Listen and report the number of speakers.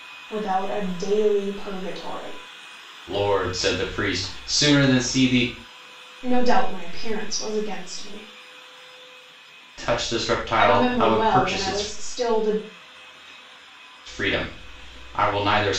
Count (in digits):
2